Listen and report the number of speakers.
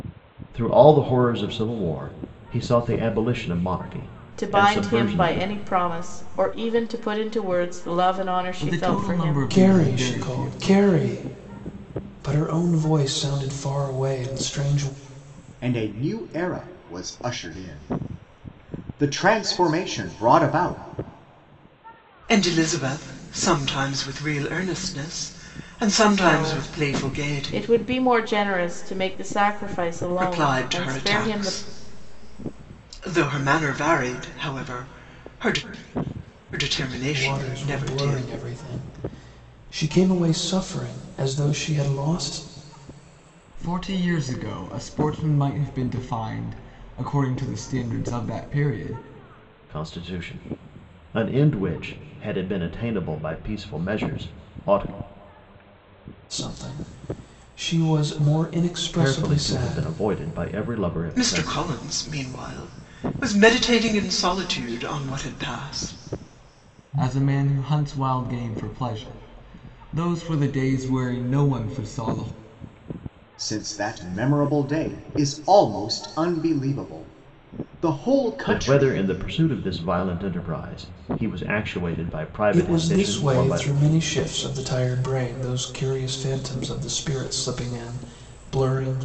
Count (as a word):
six